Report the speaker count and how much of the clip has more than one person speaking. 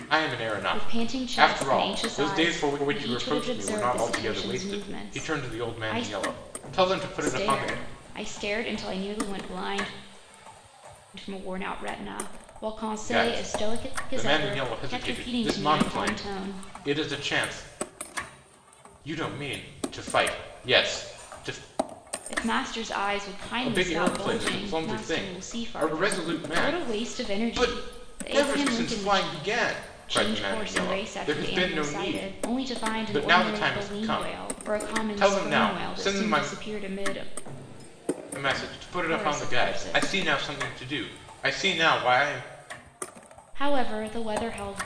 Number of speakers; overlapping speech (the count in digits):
2, about 49%